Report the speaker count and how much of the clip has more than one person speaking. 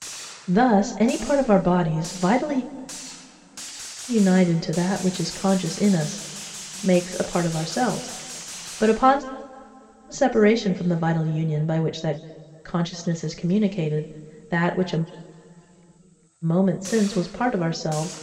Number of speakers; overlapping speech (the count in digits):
1, no overlap